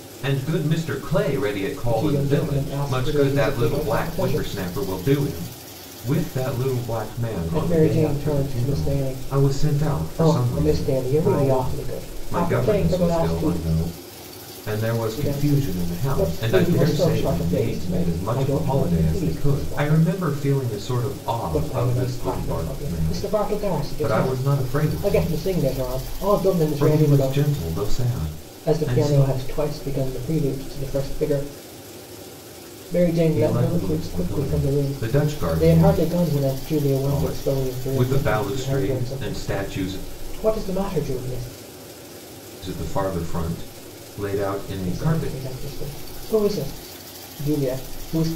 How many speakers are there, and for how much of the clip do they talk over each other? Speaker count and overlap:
2, about 50%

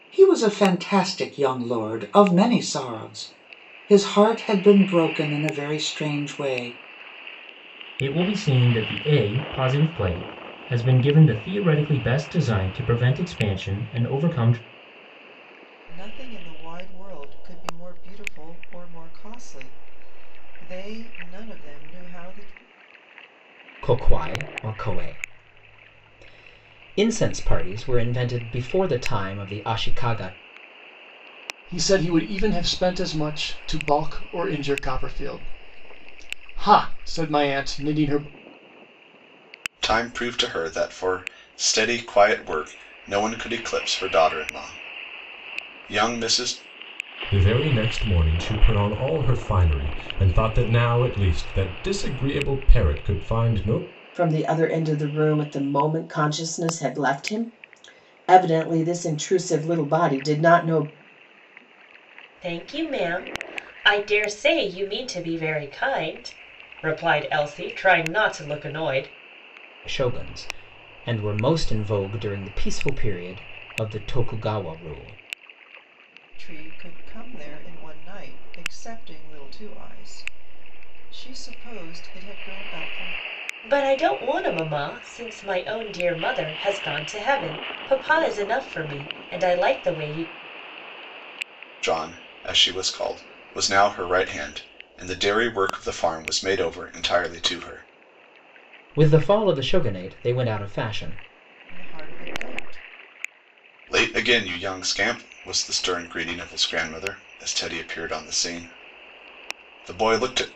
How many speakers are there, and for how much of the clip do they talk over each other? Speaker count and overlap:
9, no overlap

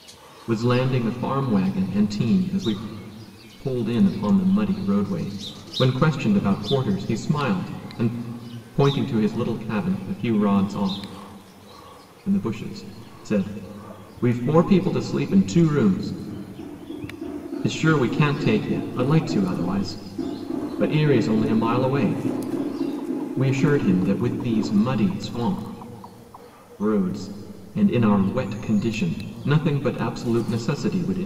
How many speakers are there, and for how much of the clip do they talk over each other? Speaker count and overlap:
1, no overlap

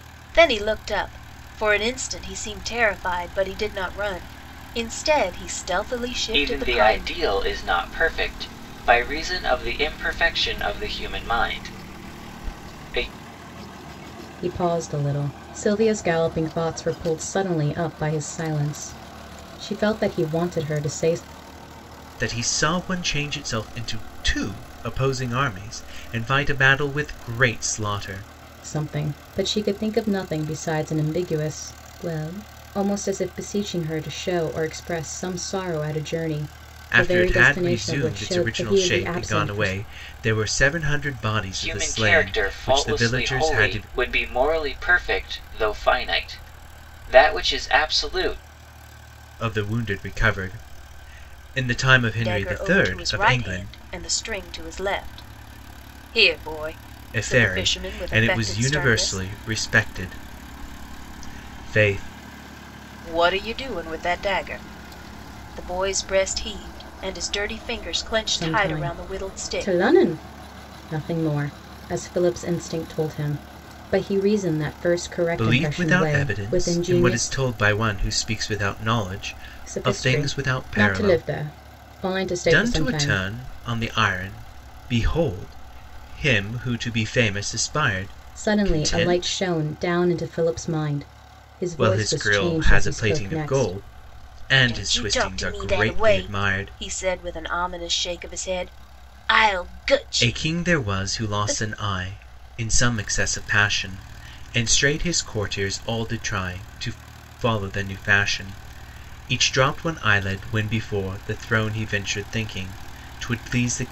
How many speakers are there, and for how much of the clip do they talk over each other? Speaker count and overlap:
4, about 20%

